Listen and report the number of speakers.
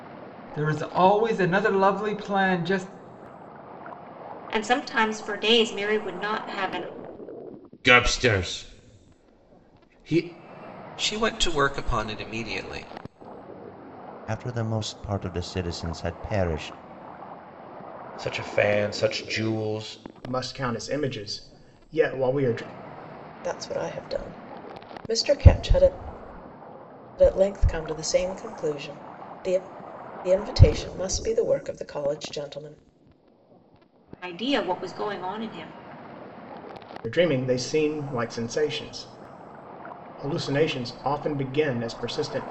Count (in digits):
8